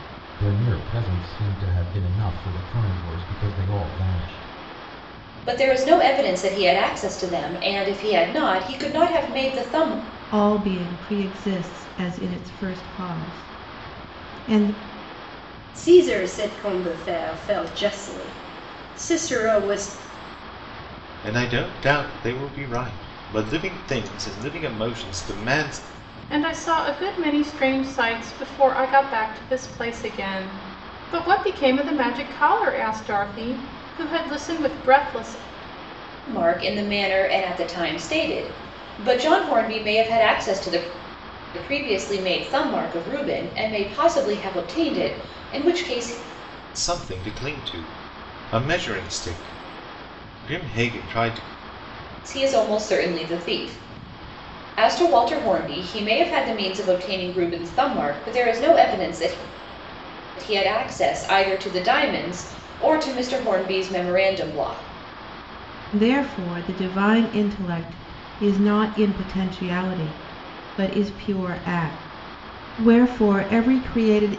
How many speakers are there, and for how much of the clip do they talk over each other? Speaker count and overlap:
6, no overlap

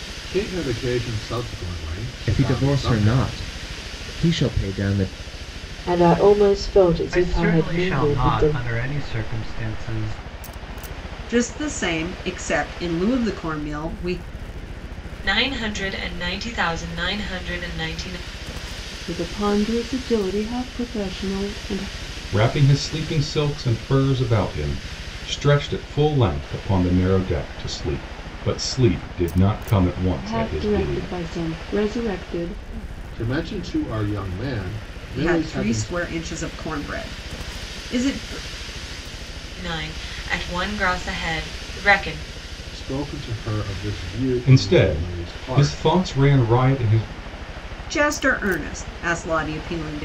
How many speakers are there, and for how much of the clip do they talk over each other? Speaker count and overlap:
8, about 11%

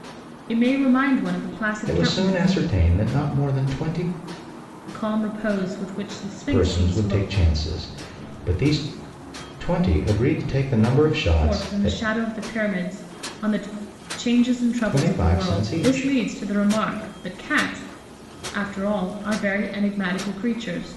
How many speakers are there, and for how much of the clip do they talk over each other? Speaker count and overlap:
2, about 18%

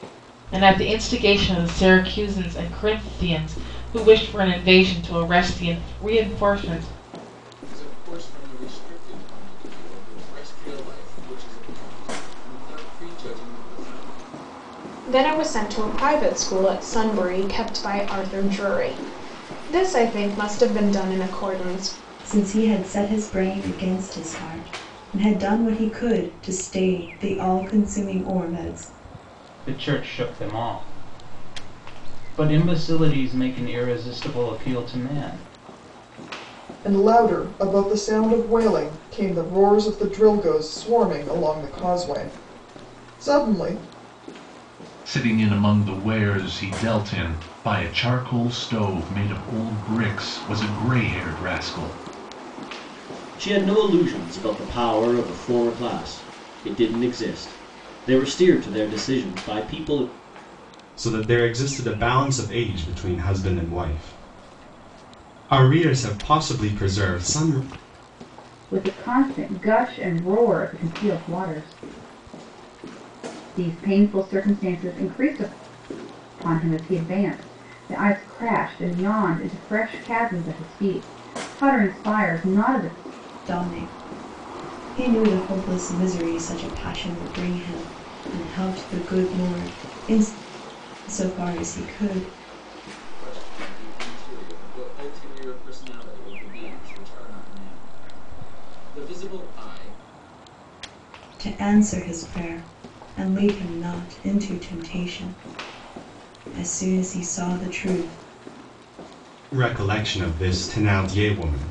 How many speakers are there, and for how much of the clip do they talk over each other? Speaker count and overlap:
10, no overlap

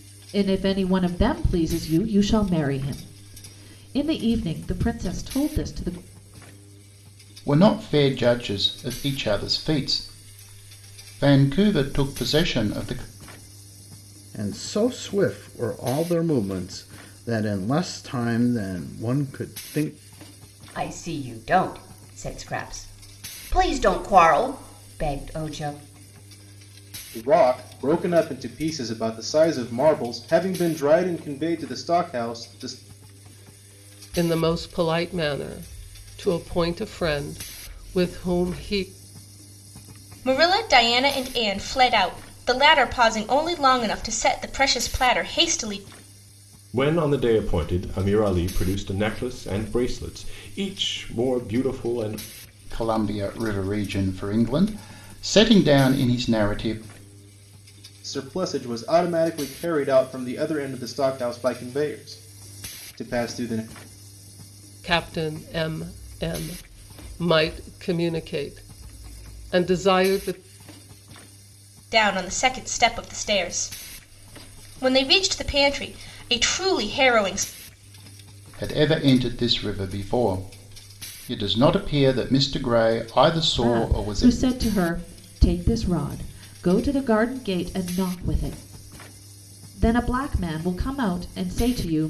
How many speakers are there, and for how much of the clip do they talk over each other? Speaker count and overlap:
8, about 1%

